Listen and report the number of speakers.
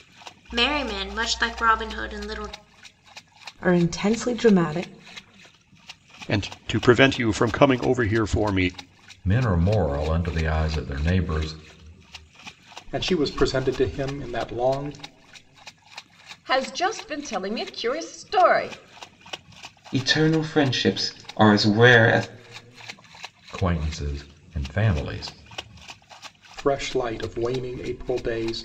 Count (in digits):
7